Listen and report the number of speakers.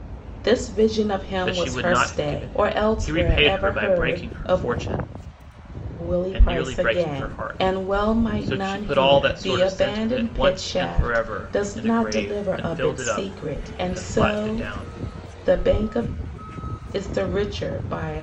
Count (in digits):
2